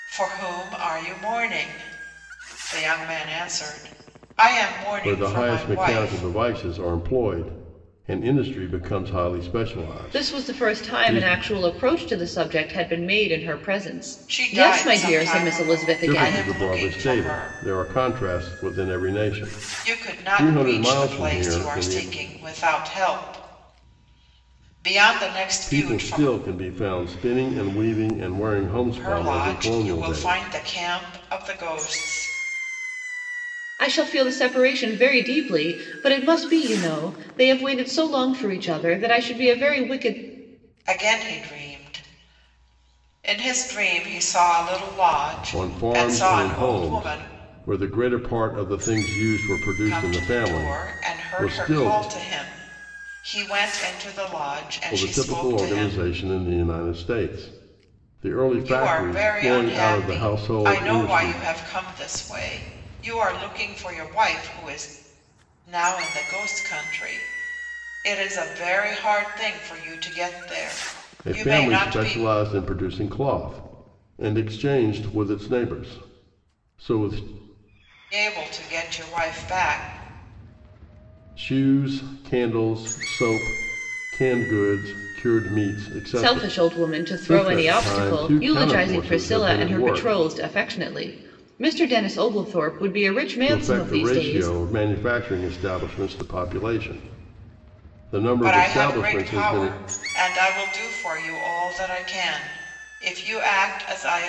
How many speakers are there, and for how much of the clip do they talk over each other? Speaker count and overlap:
3, about 25%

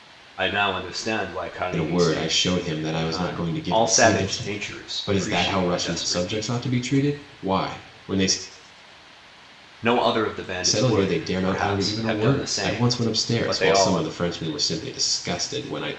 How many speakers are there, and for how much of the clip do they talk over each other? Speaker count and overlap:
2, about 49%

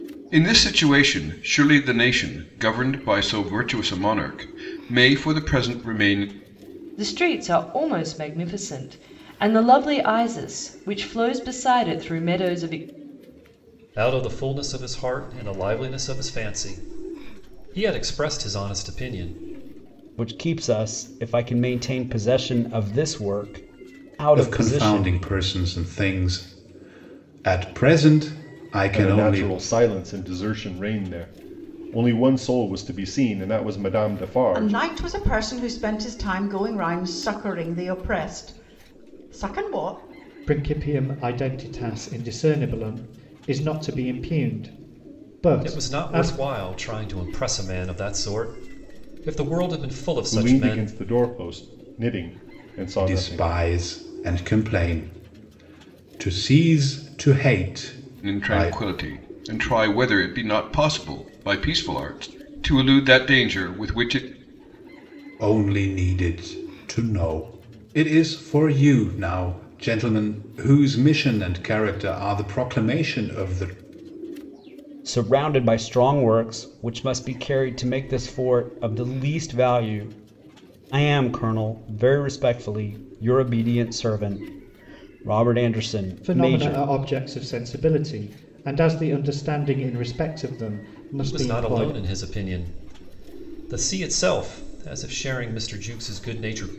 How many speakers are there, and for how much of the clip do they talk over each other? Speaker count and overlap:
8, about 6%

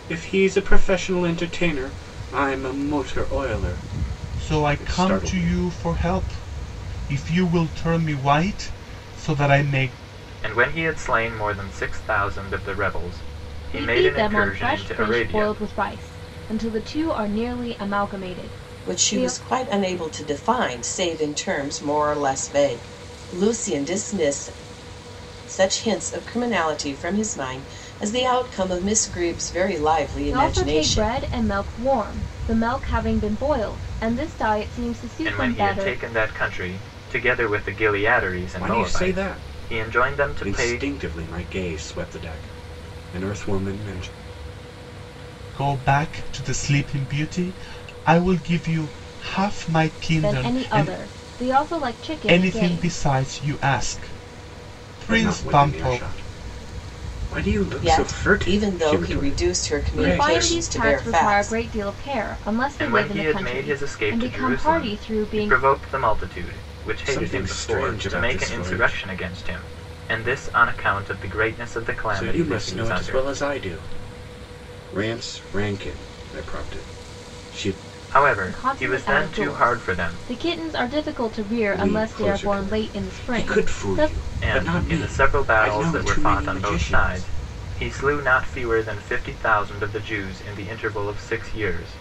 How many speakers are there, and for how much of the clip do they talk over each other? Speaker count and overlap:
5, about 29%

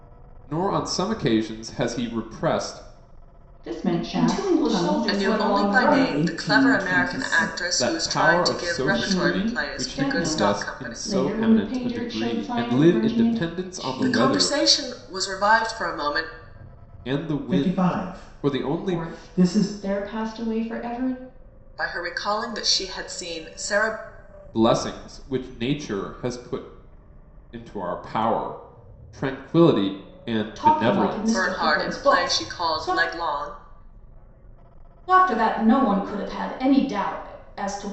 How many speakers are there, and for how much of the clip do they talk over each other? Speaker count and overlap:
5, about 40%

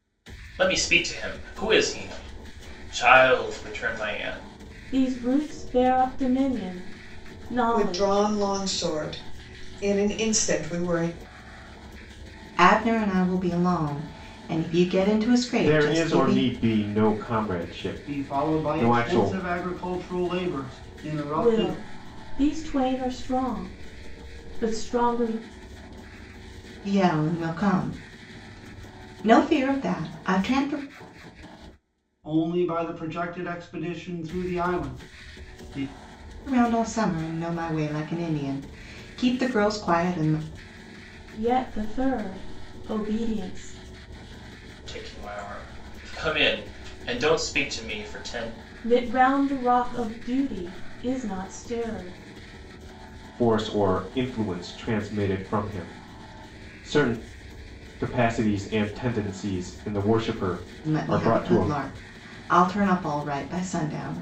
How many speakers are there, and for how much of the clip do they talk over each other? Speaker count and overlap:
6, about 6%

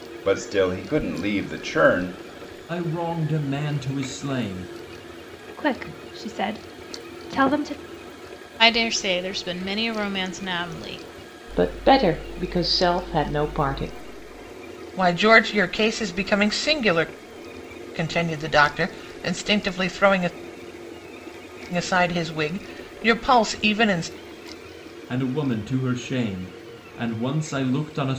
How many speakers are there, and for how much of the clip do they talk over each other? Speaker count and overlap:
6, no overlap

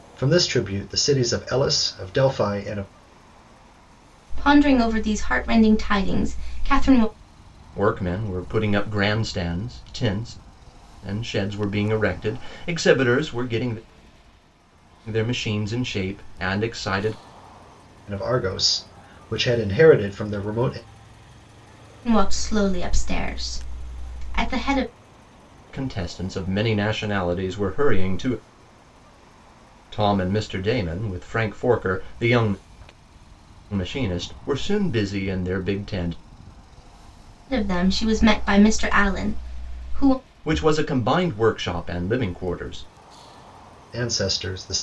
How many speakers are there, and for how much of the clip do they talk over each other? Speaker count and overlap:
3, no overlap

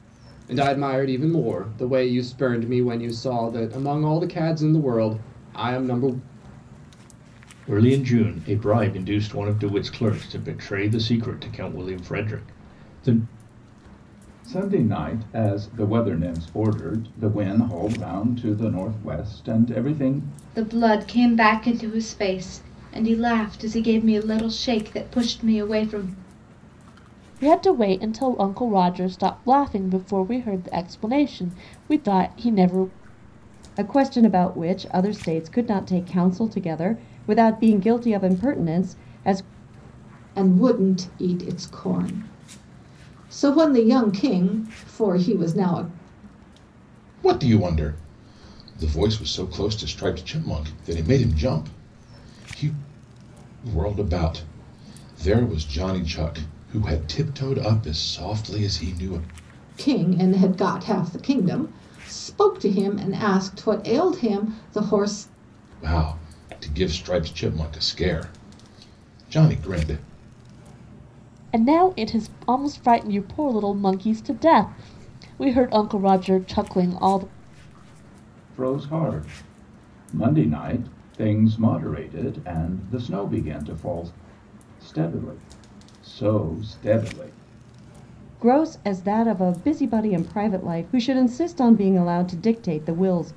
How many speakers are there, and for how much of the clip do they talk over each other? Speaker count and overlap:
8, no overlap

